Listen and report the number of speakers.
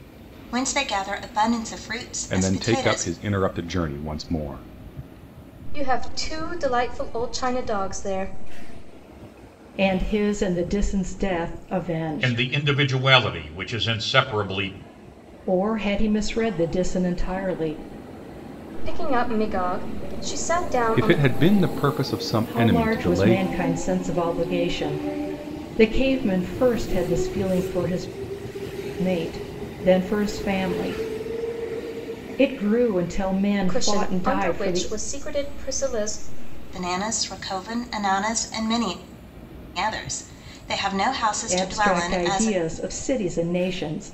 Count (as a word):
five